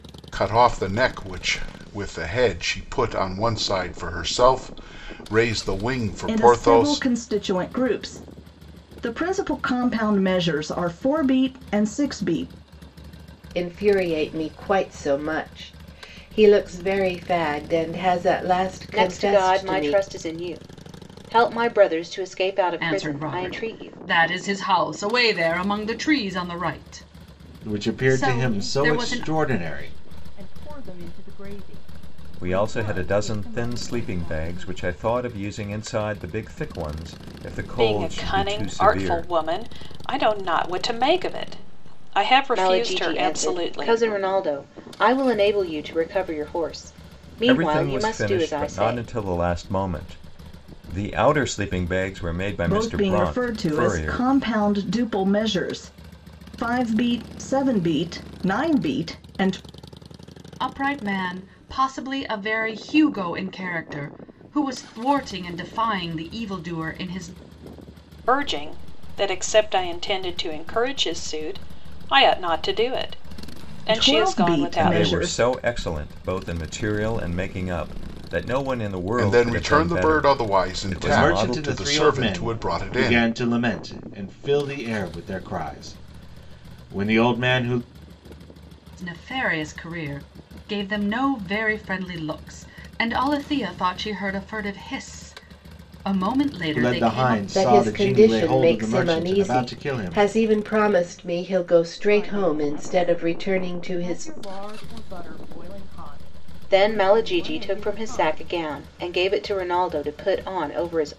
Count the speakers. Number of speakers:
9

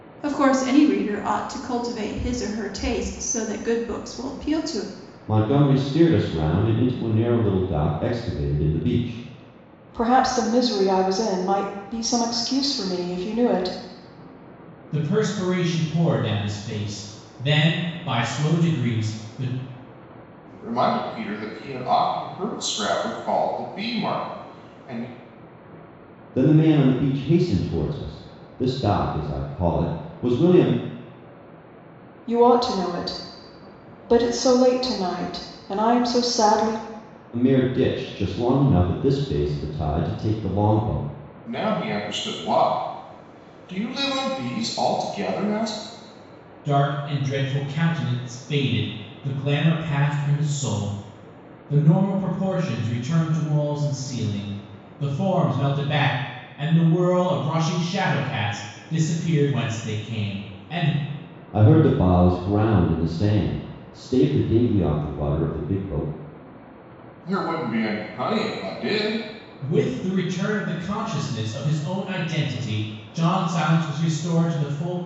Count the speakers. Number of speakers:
5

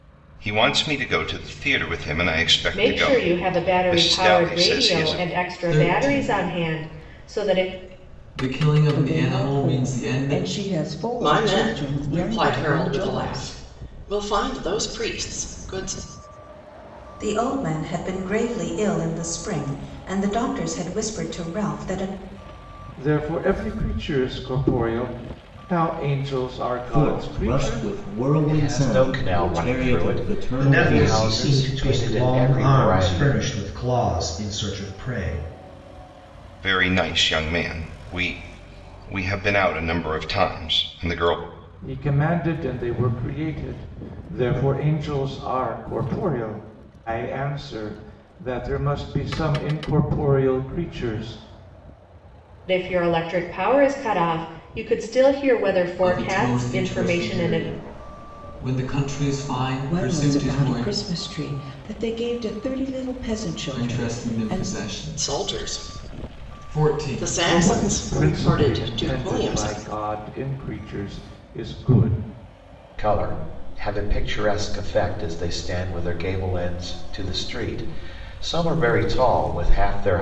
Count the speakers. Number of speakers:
10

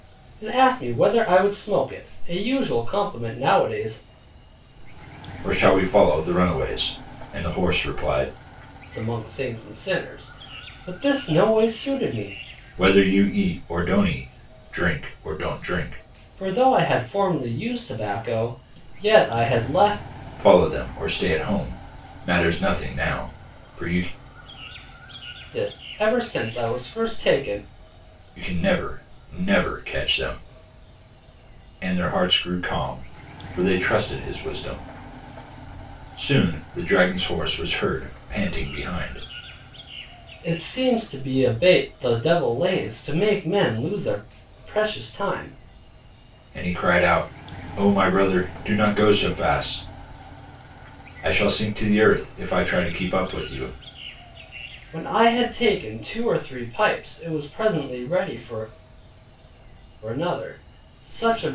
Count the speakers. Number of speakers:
2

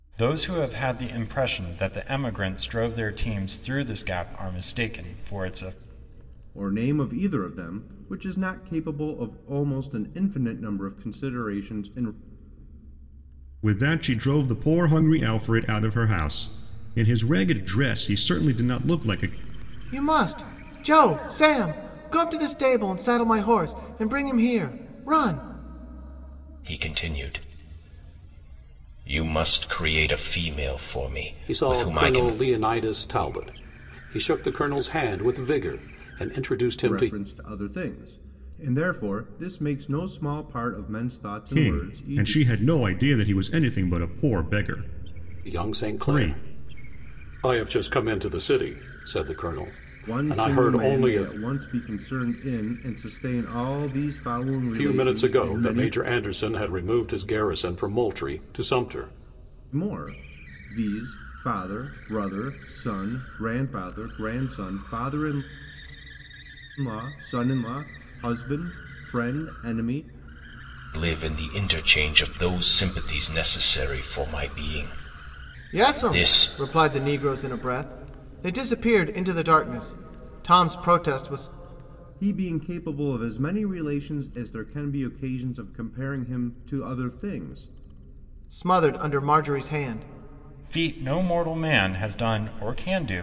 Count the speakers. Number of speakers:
6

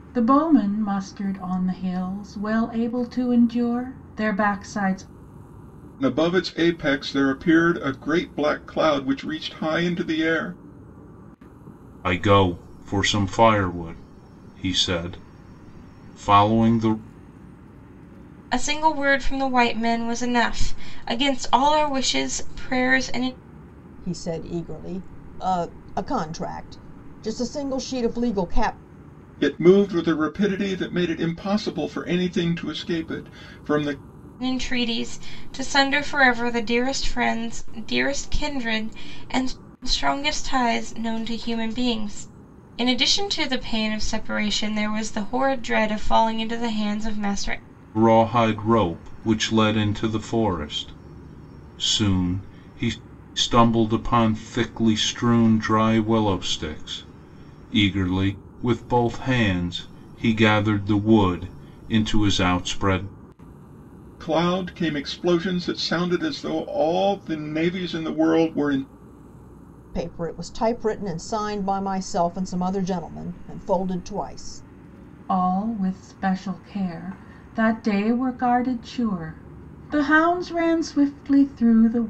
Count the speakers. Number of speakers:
5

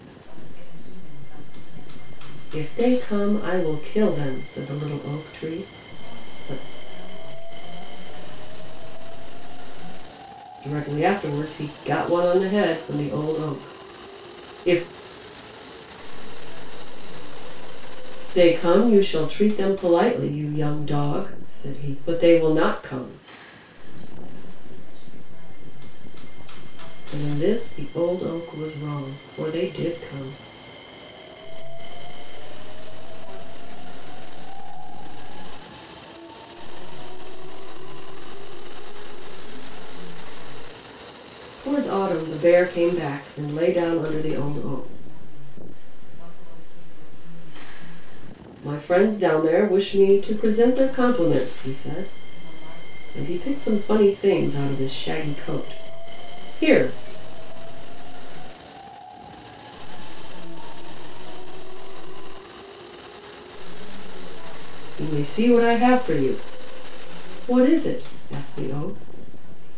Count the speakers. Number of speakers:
2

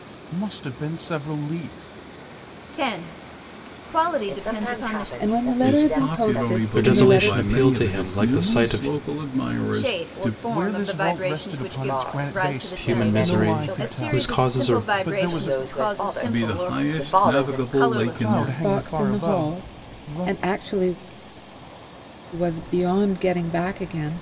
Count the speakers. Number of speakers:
6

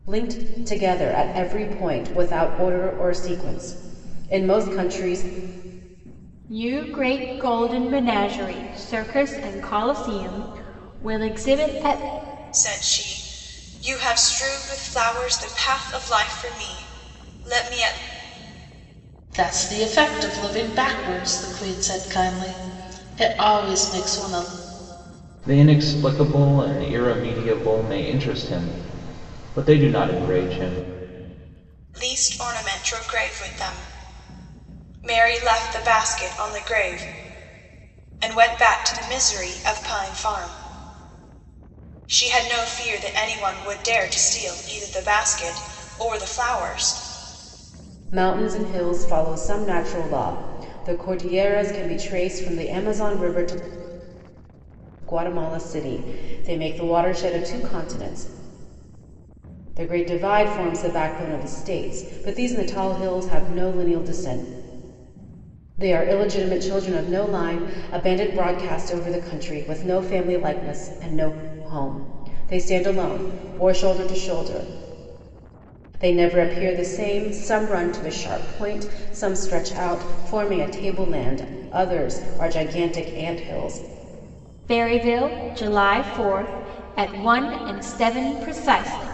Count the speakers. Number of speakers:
5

